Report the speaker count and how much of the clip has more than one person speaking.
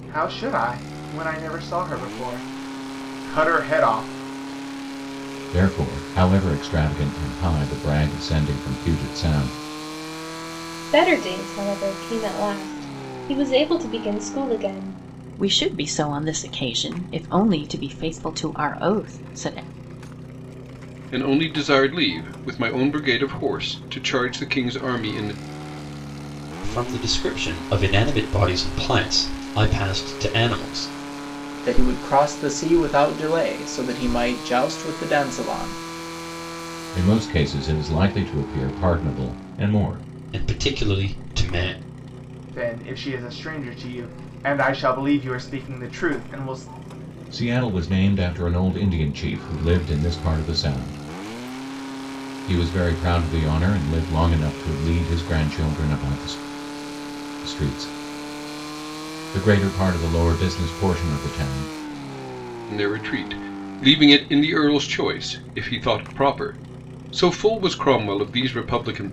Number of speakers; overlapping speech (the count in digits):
7, no overlap